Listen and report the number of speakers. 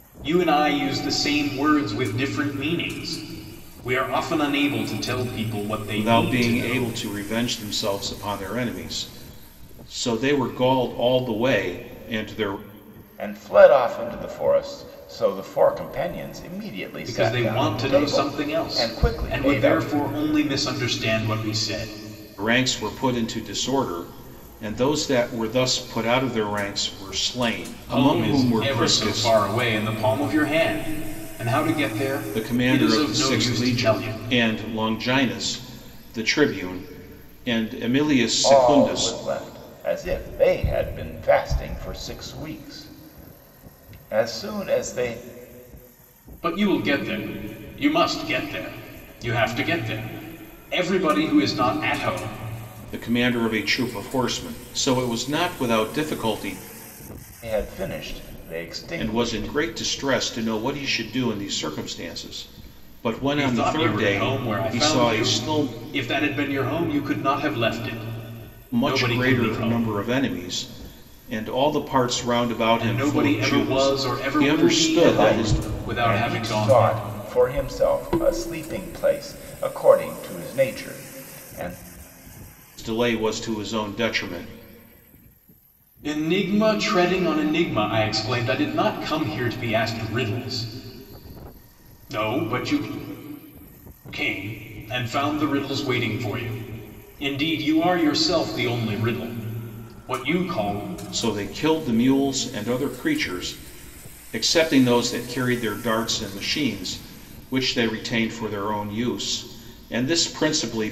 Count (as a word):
three